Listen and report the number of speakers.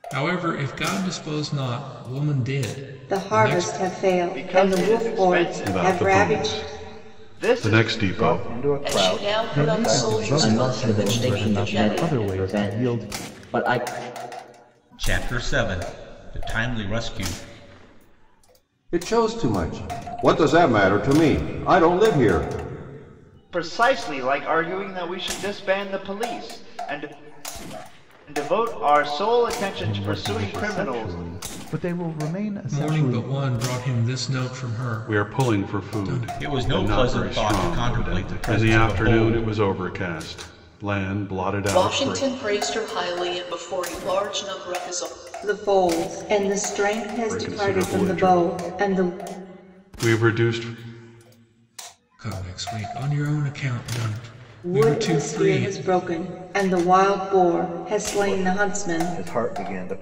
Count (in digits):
10